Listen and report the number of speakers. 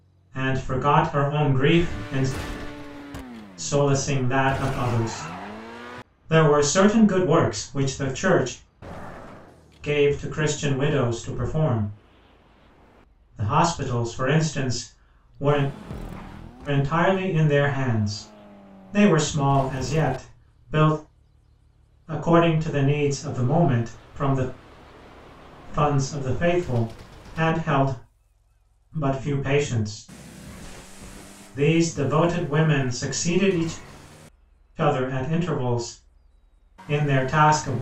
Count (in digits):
1